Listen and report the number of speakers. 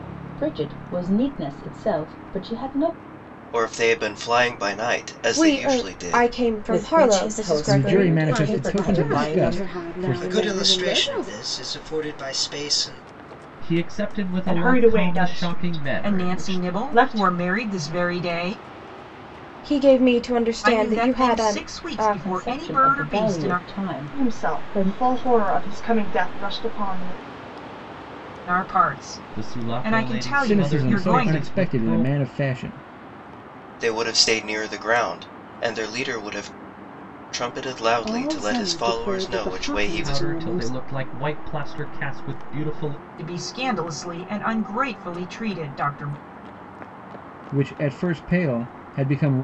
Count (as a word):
ten